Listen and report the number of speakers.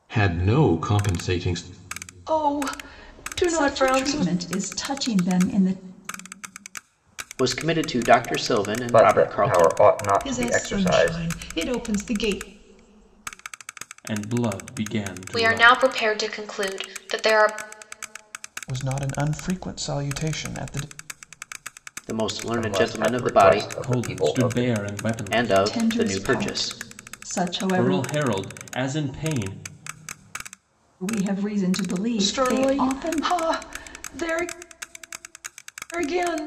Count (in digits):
9